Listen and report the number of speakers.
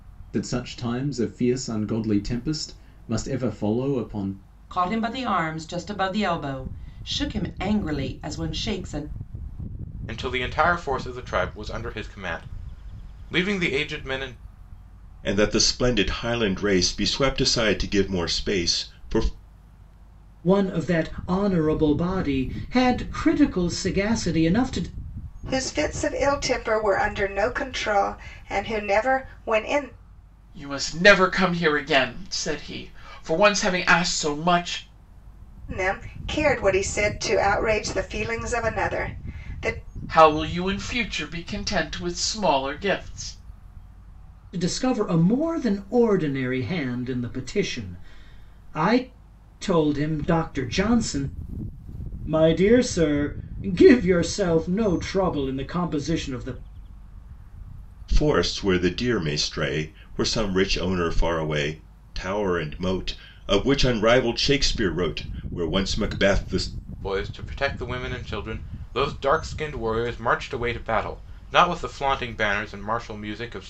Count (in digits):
7